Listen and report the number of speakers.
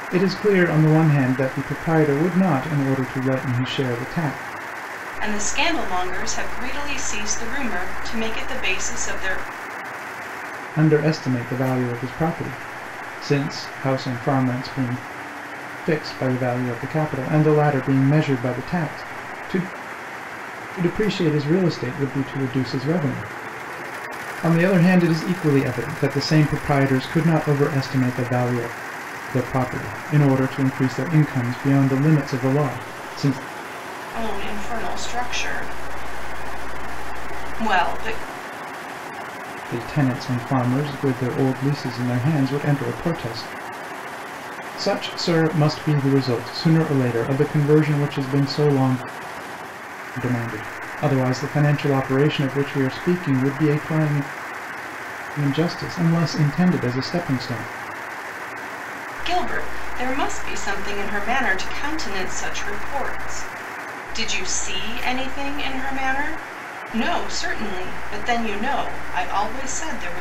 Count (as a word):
two